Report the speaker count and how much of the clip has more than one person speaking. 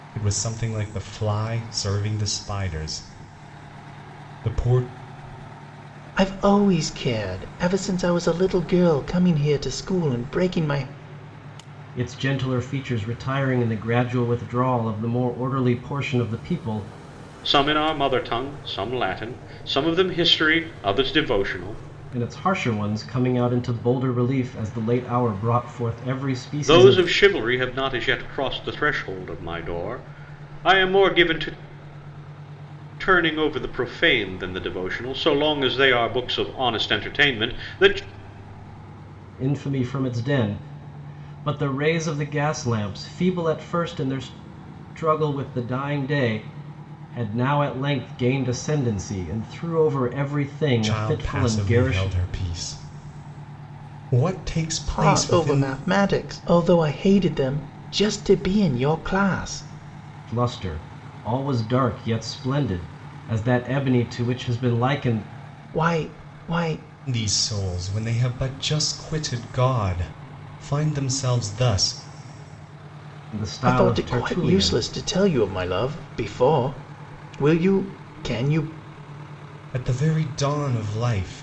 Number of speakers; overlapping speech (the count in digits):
4, about 5%